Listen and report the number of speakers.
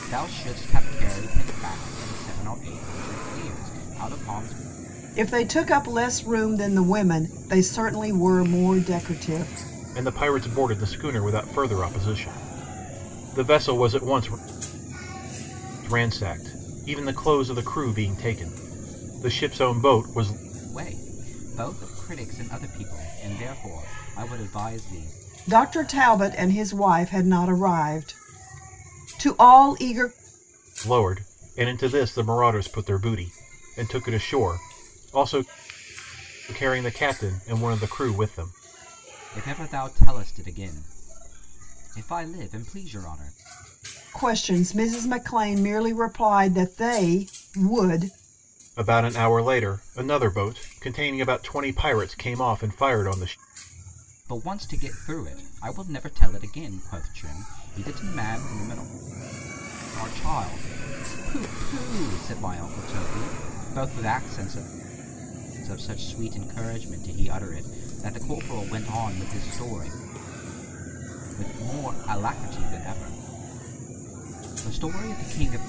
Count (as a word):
three